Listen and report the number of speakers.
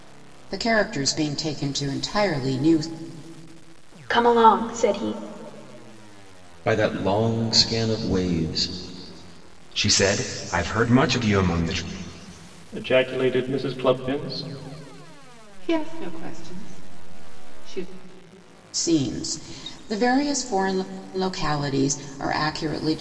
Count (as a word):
six